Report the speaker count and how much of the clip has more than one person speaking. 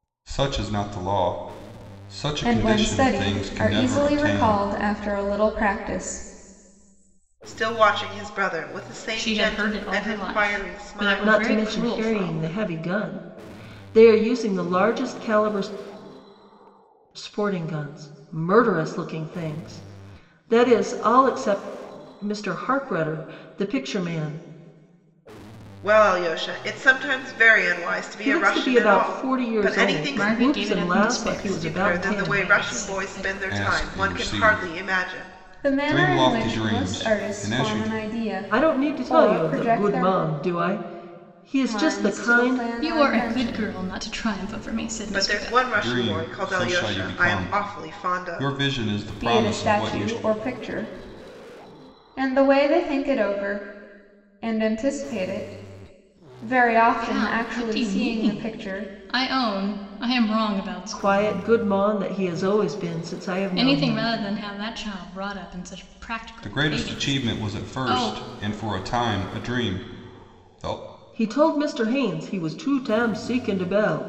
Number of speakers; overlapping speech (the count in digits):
5, about 38%